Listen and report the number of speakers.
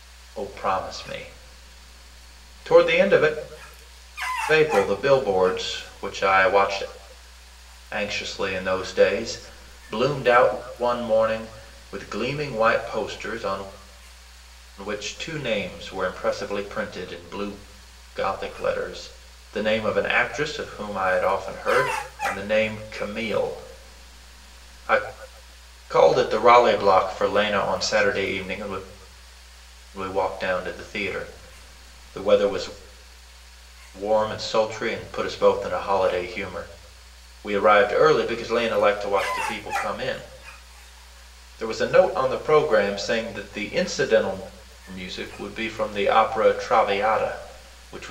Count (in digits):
1